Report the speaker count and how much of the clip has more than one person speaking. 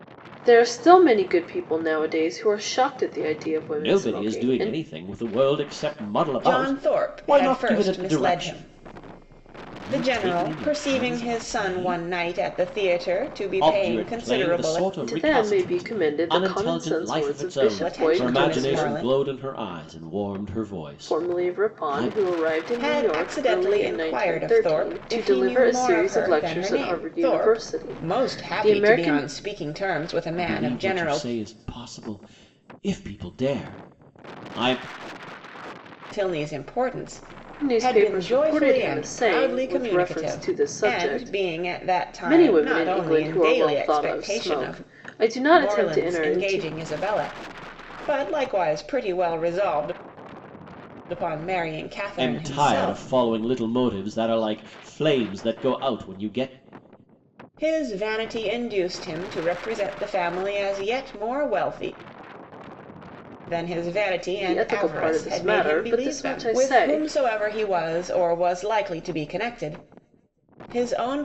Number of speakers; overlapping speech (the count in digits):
3, about 44%